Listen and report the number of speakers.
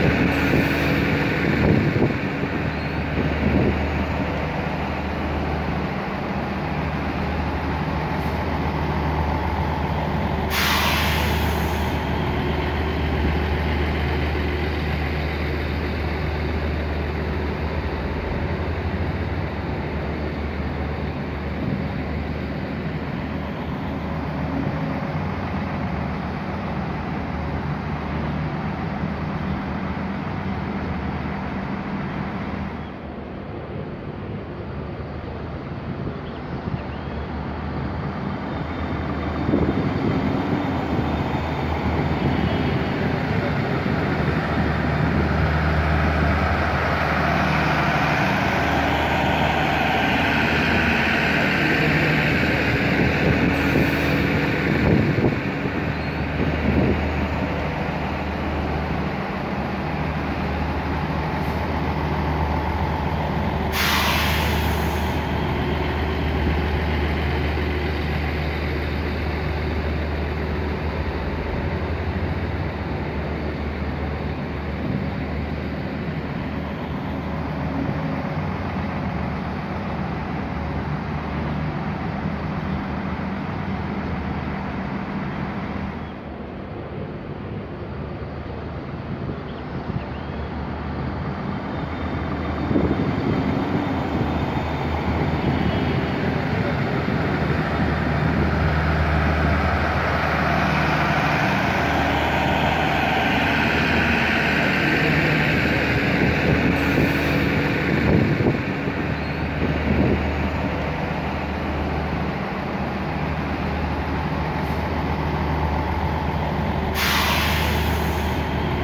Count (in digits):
0